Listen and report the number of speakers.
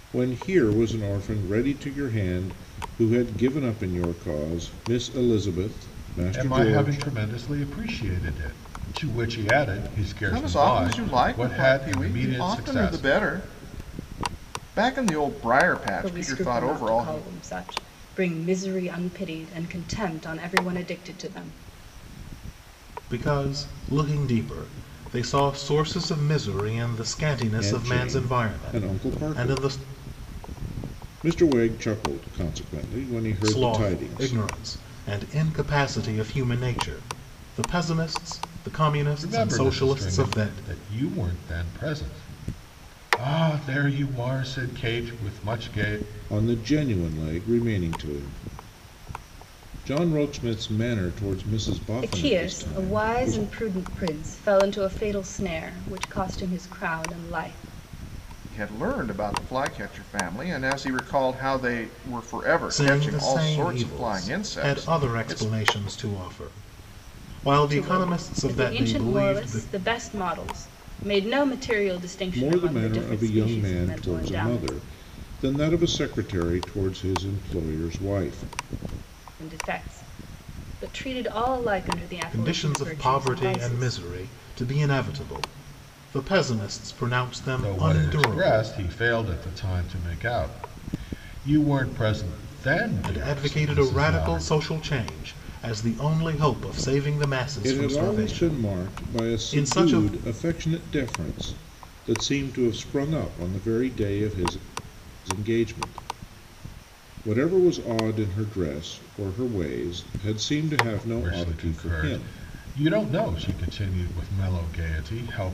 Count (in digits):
5